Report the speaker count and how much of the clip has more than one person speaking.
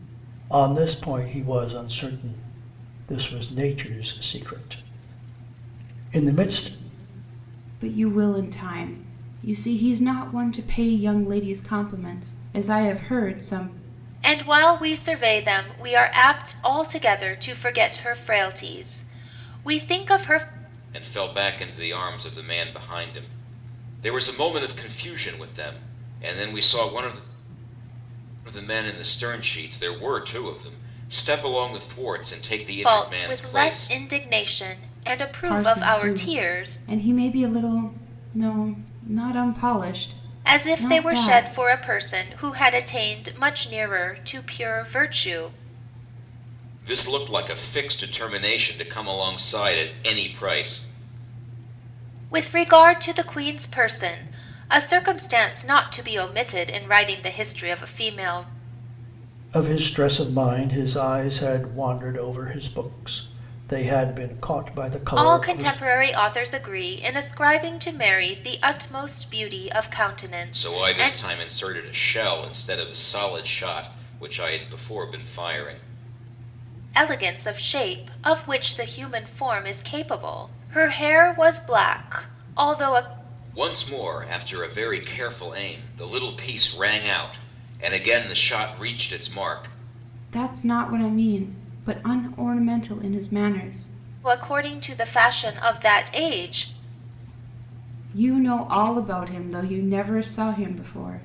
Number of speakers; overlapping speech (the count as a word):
four, about 5%